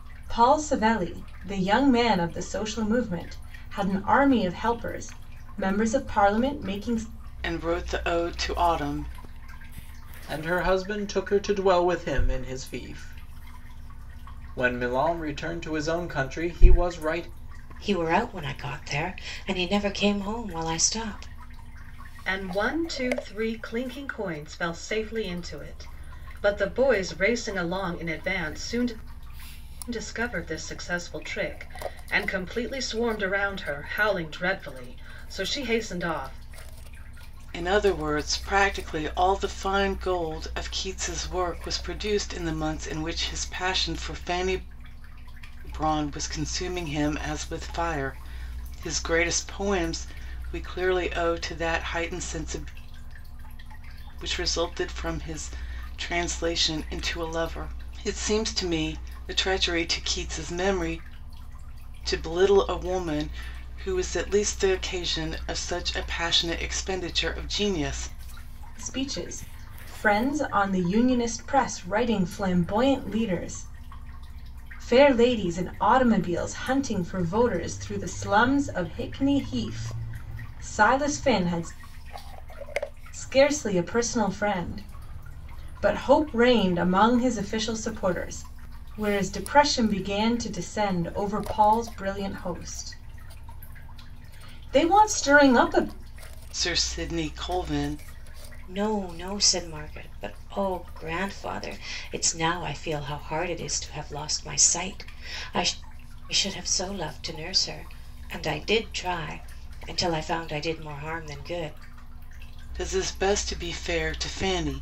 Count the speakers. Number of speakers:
five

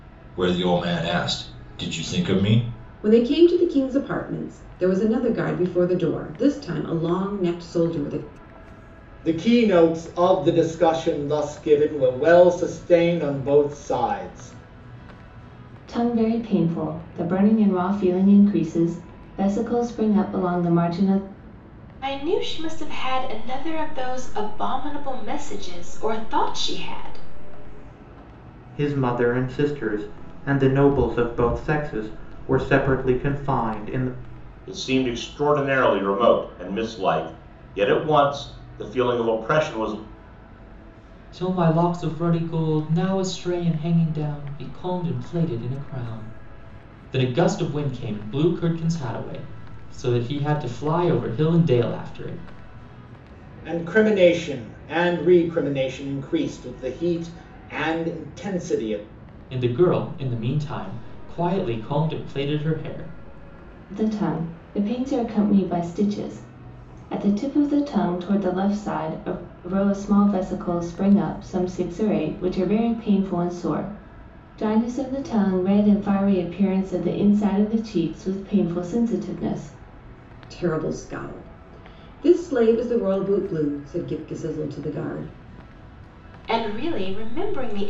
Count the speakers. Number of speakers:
eight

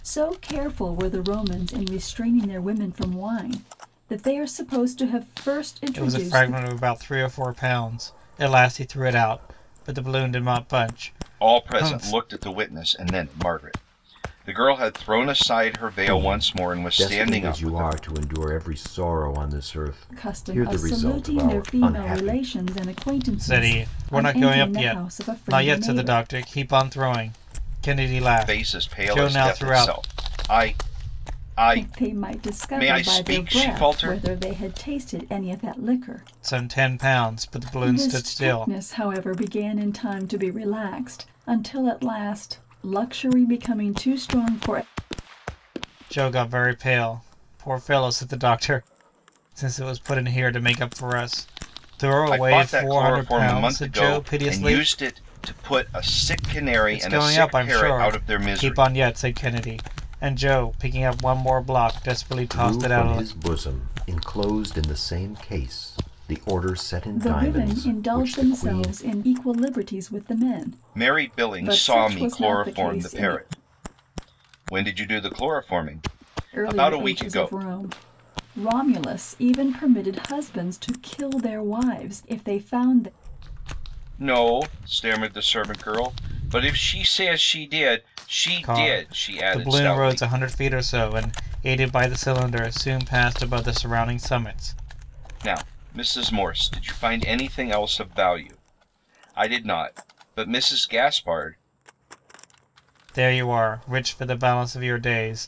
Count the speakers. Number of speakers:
four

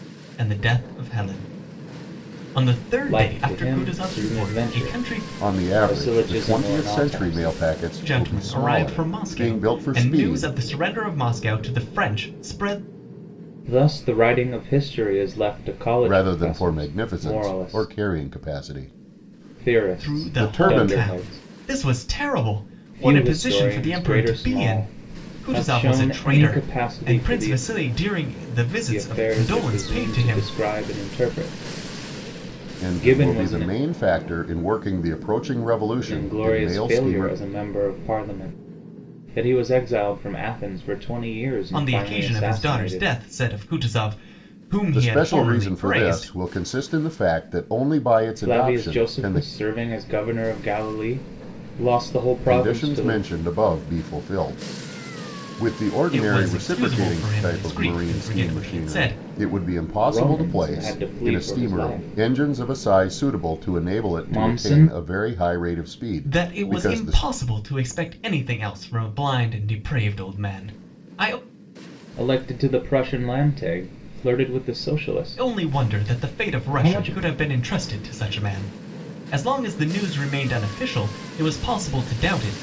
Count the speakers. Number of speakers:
three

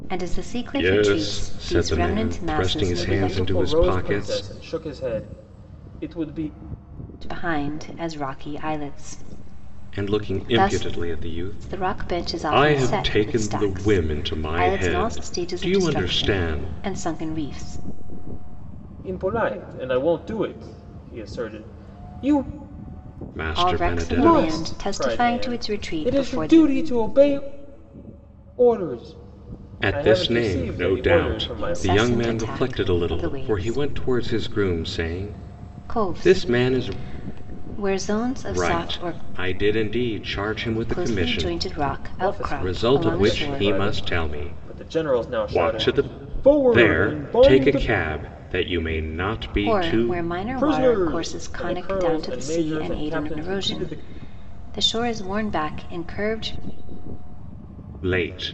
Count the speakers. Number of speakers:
three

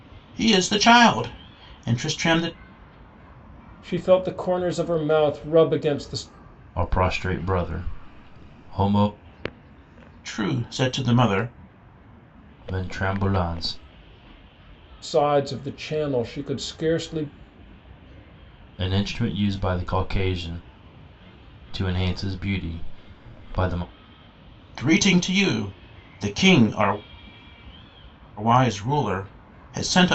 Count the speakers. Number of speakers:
three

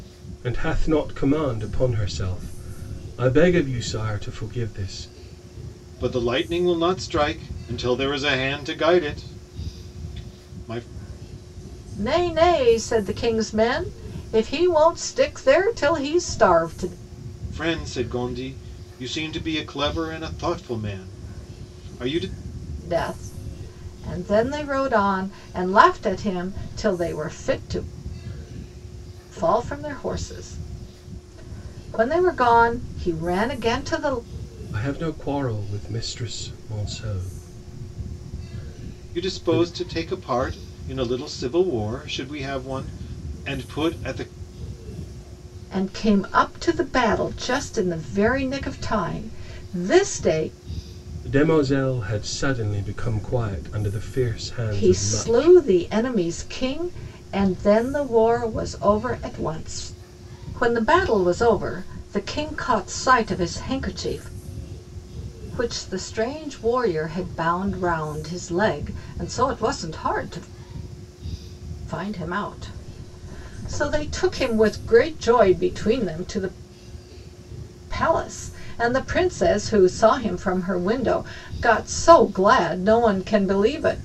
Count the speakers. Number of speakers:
three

